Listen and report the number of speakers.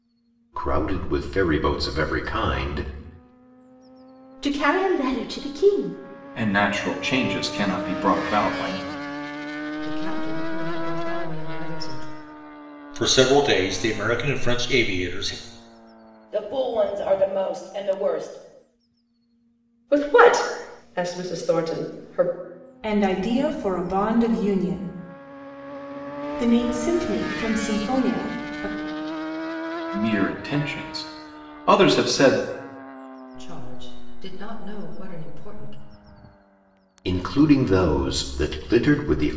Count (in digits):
8